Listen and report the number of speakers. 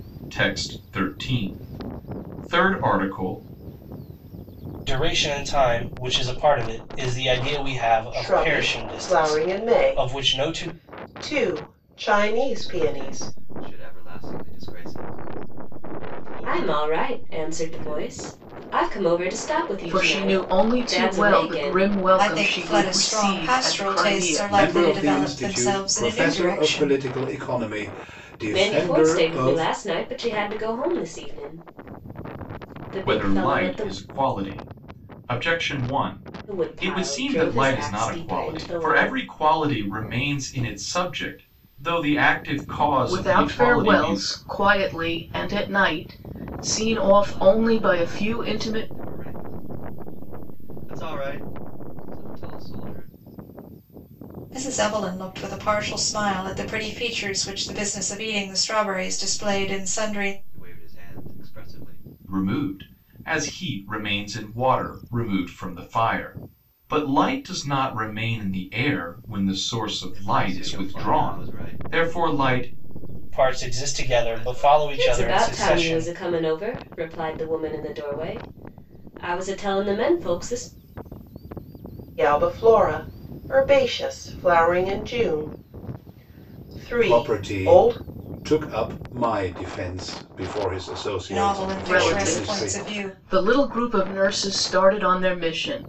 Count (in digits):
8